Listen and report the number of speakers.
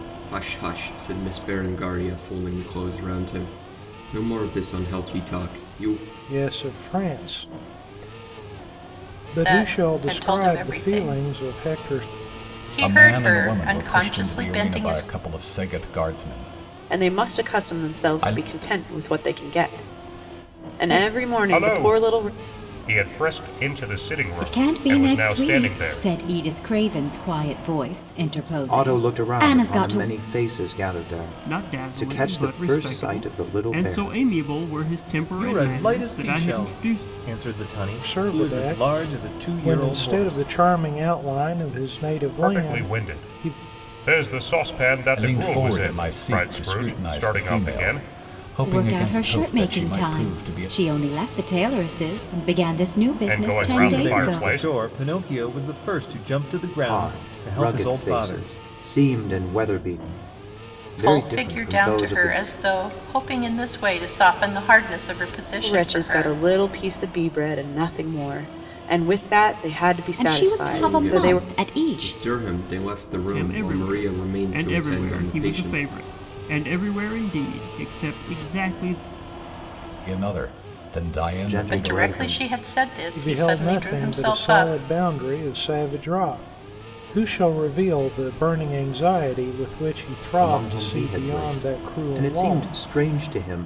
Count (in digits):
10